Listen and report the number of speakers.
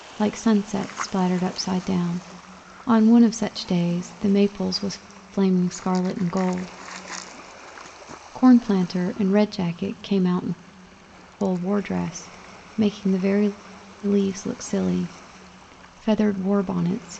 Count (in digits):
1